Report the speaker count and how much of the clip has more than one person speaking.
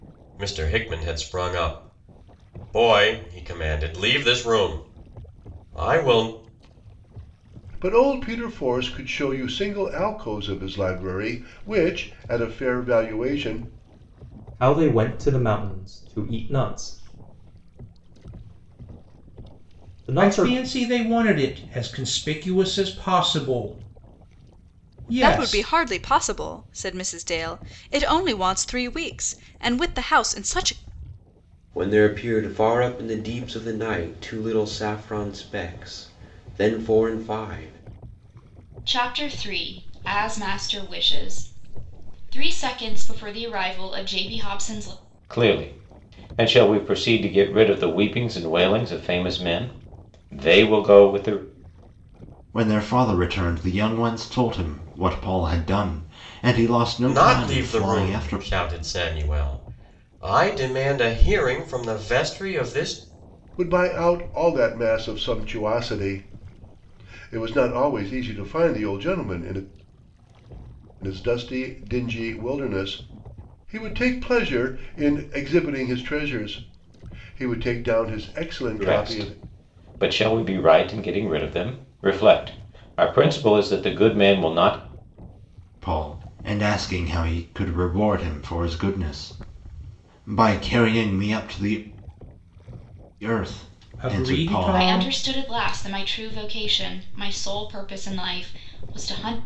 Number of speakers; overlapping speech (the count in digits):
9, about 4%